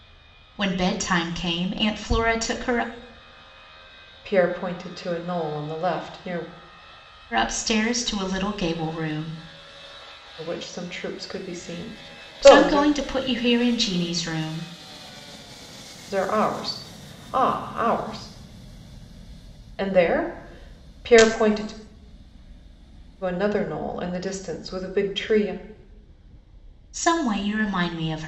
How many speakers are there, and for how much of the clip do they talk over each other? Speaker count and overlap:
two, about 2%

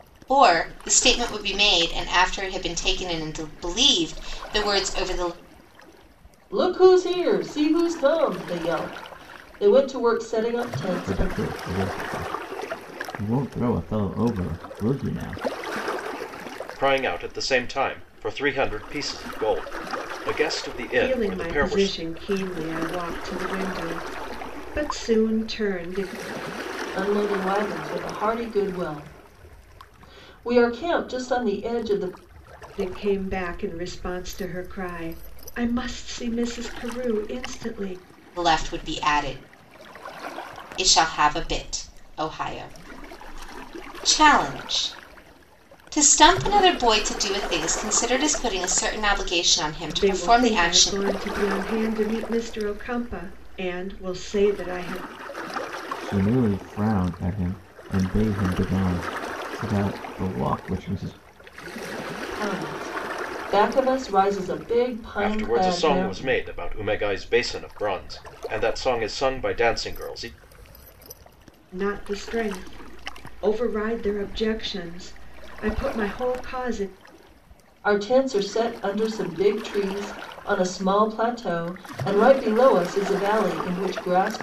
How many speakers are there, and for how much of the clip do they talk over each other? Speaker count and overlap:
five, about 4%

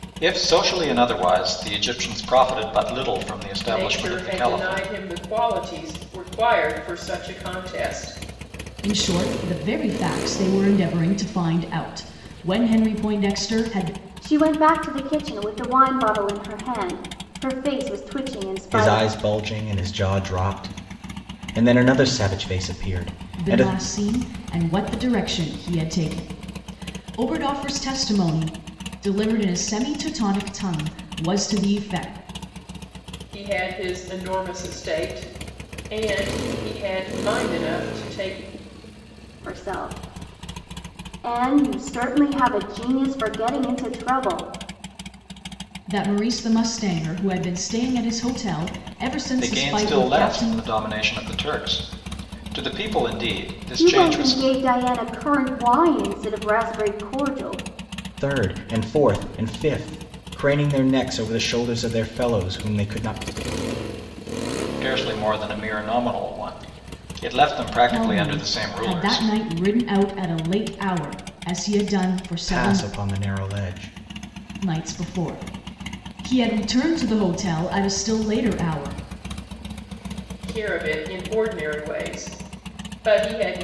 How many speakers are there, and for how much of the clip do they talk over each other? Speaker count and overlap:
five, about 7%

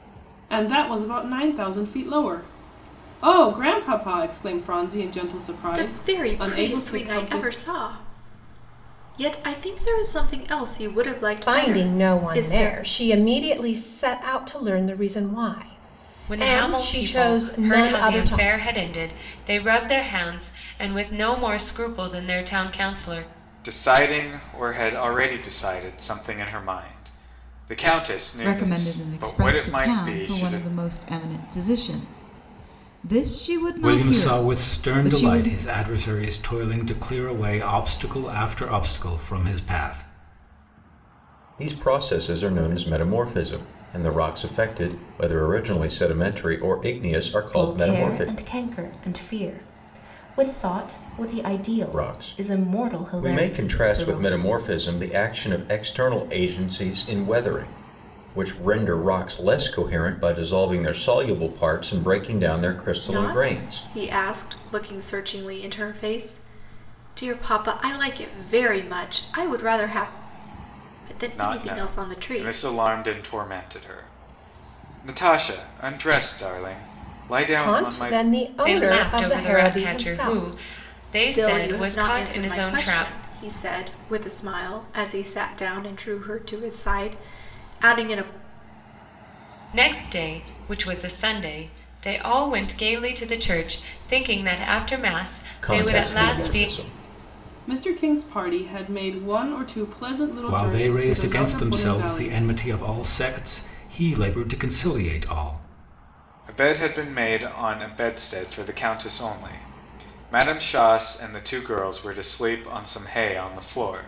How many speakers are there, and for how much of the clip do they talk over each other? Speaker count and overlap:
nine, about 21%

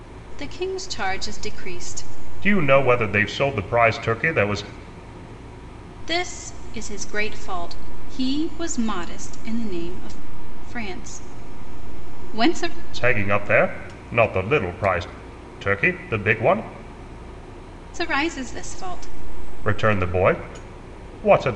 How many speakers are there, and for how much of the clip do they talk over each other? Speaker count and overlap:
two, no overlap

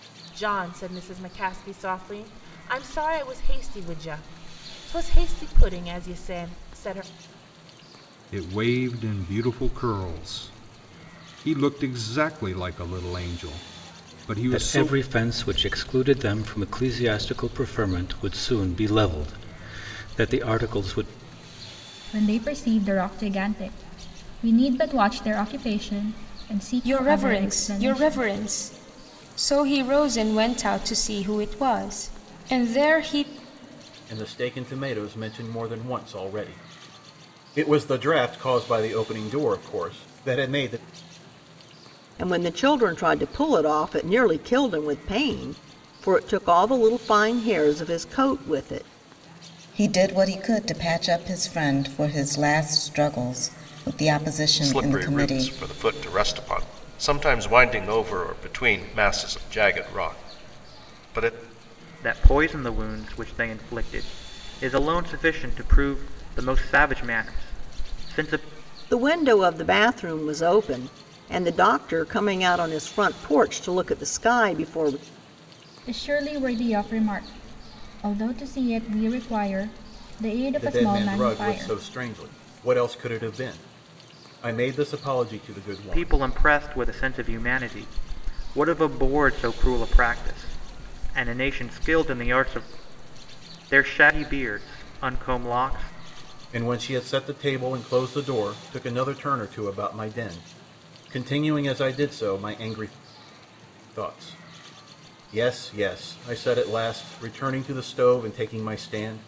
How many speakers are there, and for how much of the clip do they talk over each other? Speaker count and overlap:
ten, about 4%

